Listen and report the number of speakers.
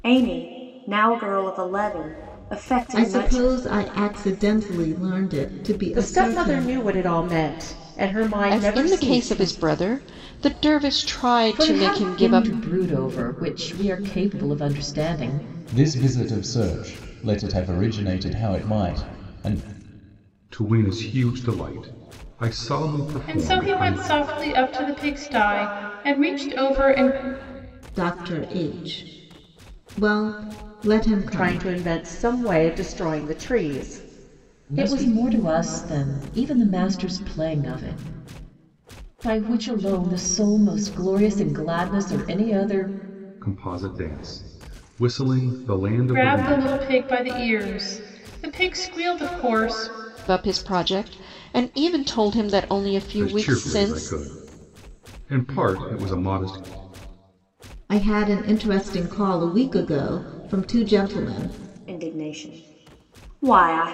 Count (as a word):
eight